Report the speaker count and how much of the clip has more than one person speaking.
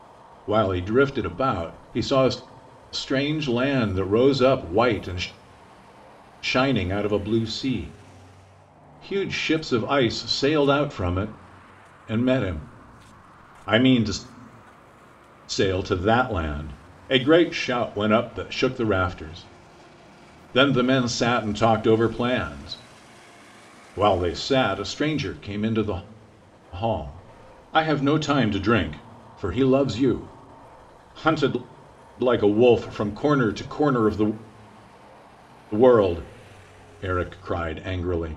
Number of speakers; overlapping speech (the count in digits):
1, no overlap